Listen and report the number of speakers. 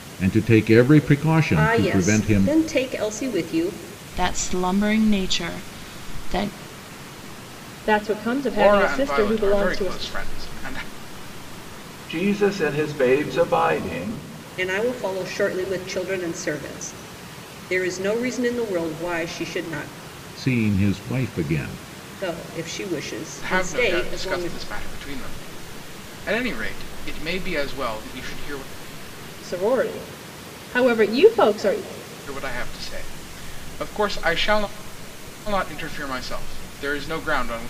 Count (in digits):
6